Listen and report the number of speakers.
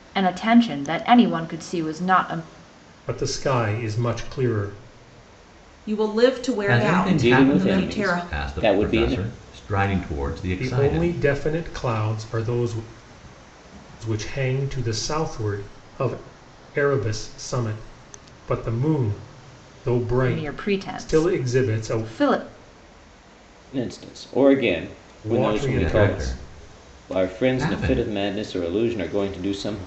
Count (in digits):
5